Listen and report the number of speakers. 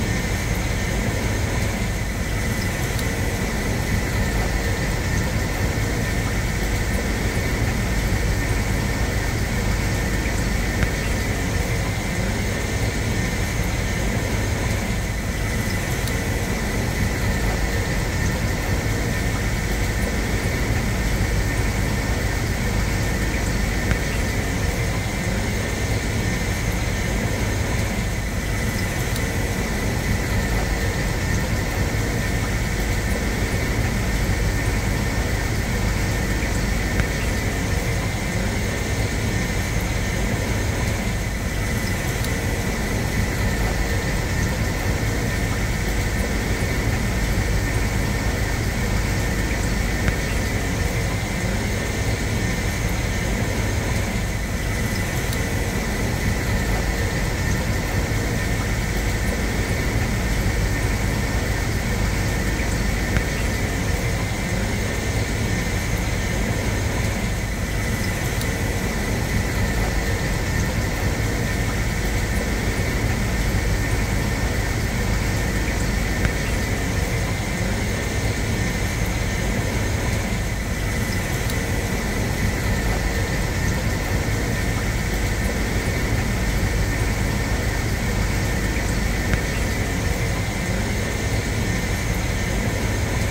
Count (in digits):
0